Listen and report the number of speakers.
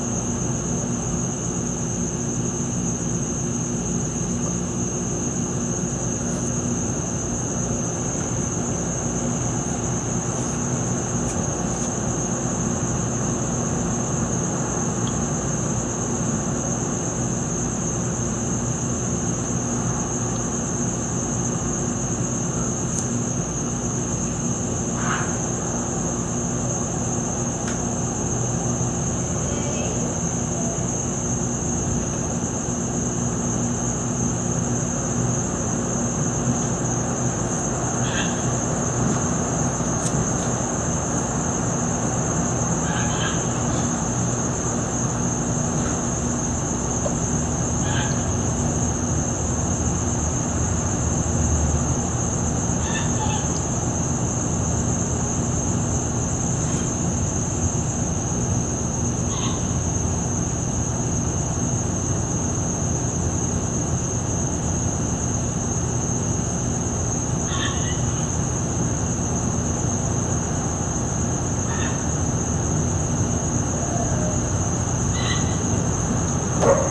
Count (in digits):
0